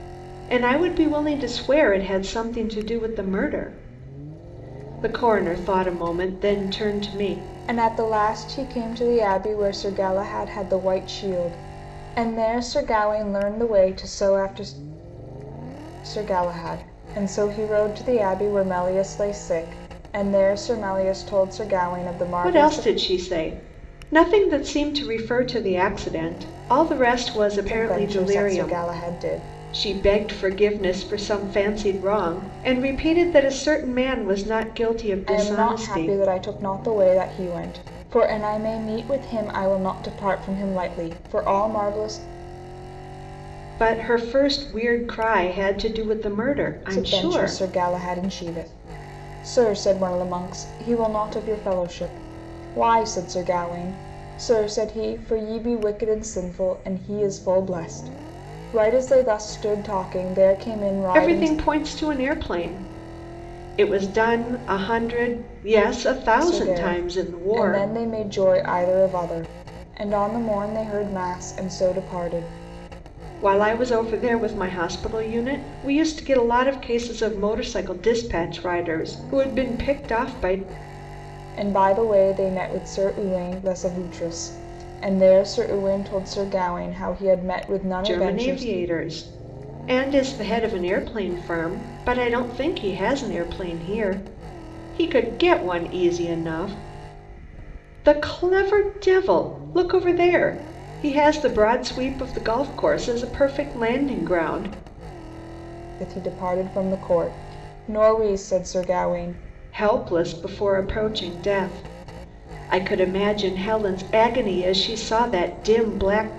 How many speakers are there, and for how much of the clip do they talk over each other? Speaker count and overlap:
2, about 5%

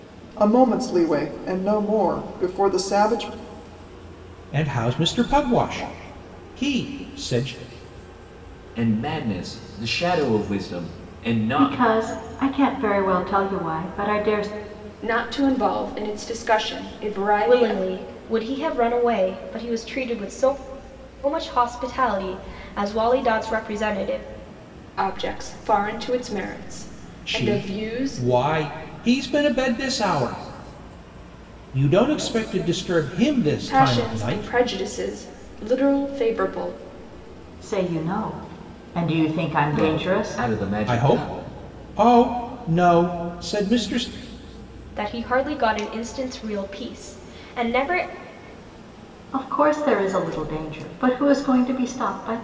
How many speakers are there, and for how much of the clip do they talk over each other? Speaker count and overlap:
6, about 8%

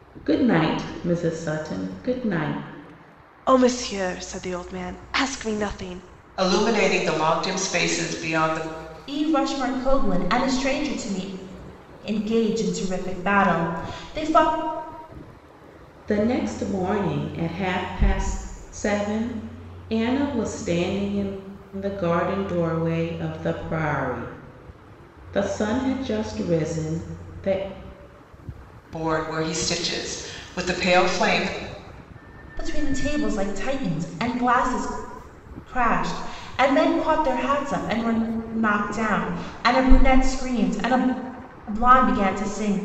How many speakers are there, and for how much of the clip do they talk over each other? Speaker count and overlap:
4, no overlap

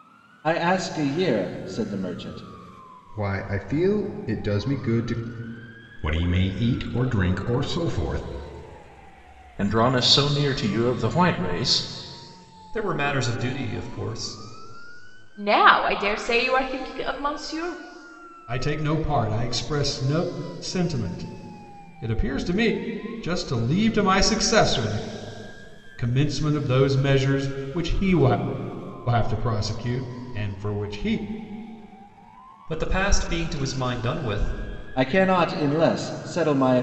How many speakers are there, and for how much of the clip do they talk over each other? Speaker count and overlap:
7, no overlap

